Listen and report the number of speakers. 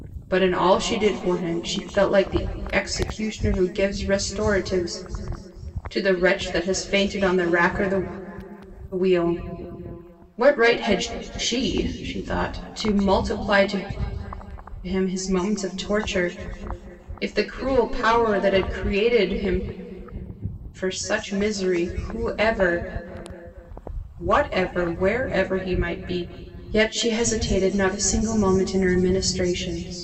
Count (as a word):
one